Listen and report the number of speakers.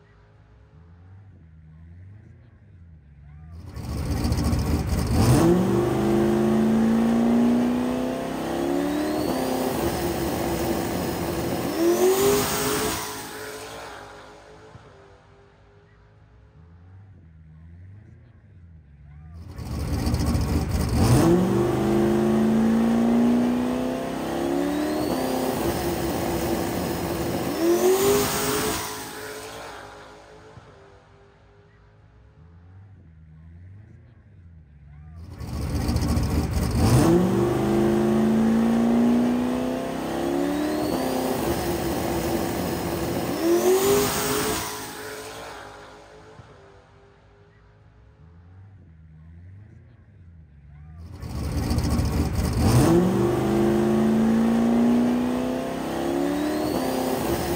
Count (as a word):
zero